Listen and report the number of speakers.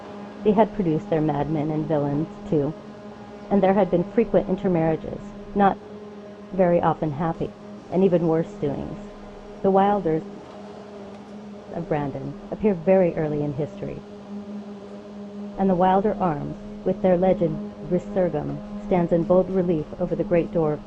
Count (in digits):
1